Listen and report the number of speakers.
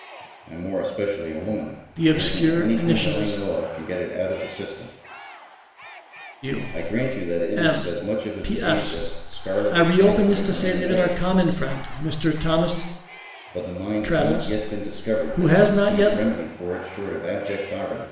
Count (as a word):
two